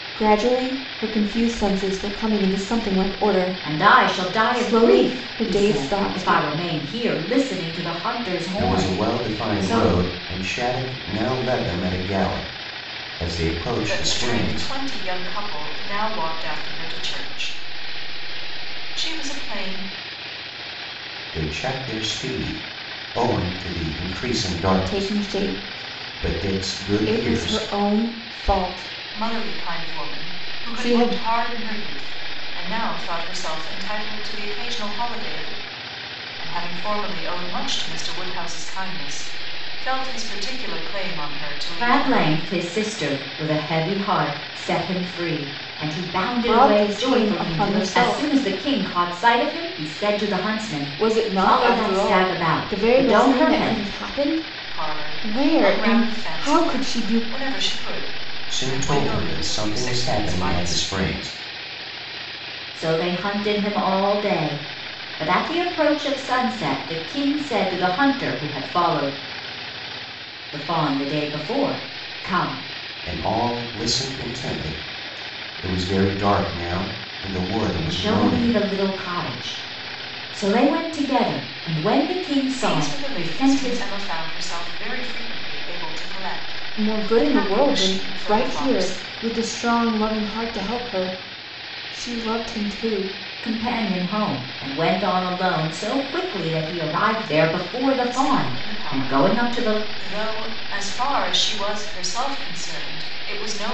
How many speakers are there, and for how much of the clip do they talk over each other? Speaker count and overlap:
four, about 26%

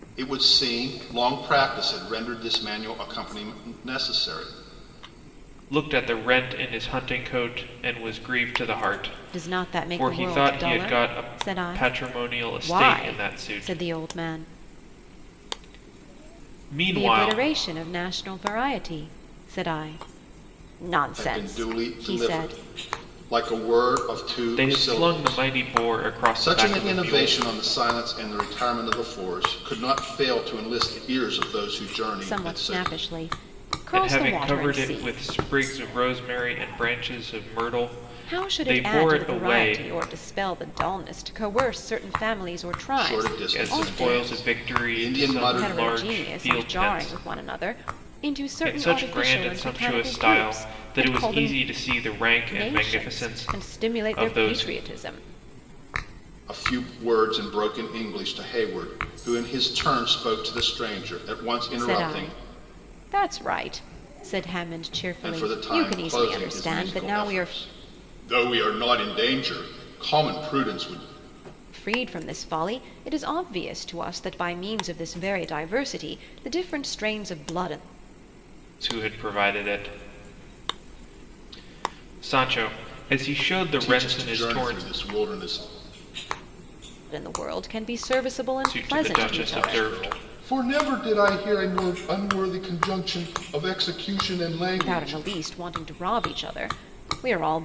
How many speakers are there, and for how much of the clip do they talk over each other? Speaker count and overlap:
three, about 29%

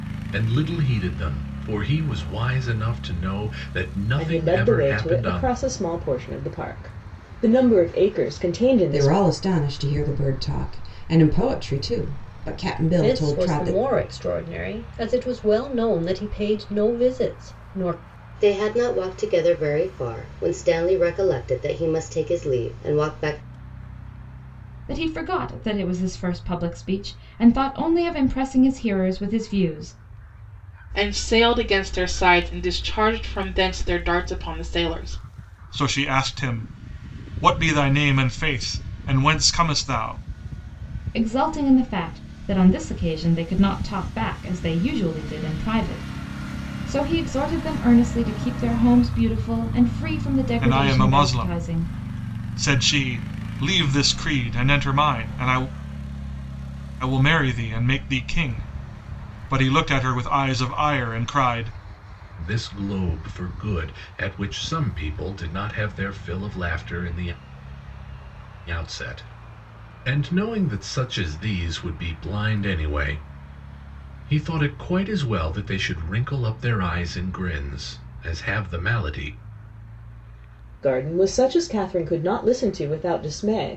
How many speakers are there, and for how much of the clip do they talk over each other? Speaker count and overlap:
eight, about 5%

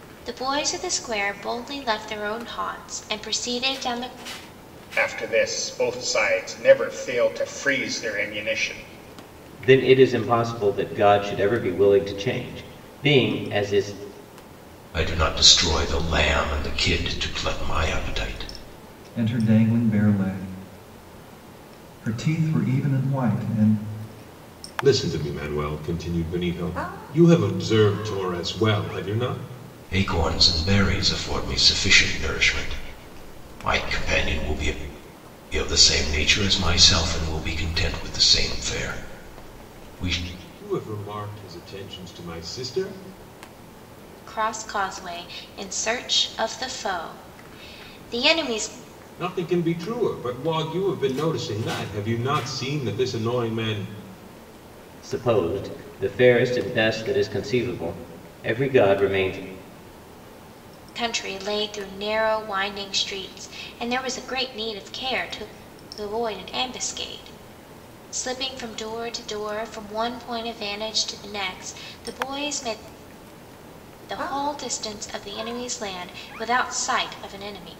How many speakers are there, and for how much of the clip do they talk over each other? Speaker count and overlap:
six, no overlap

